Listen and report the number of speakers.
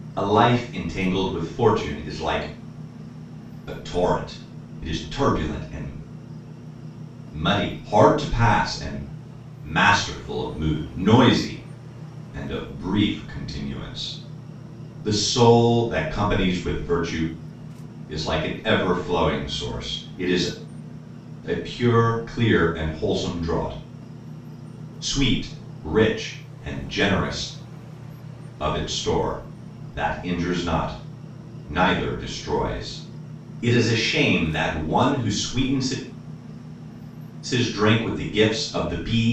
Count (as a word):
one